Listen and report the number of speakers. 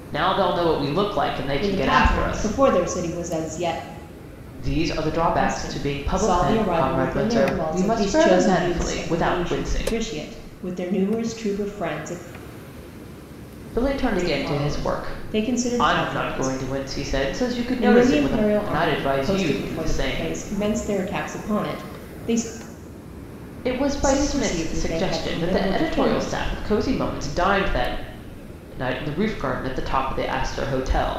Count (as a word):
two